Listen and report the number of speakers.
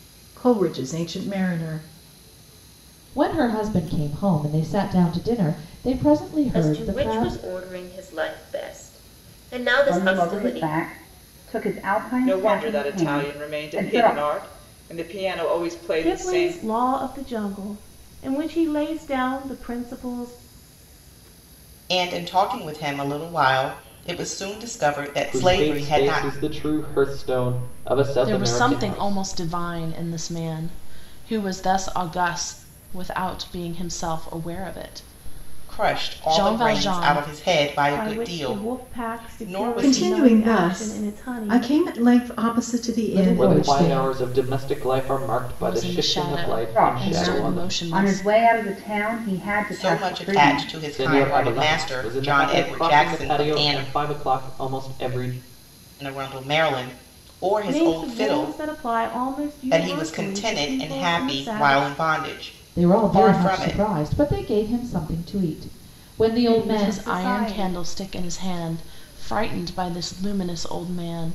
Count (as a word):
nine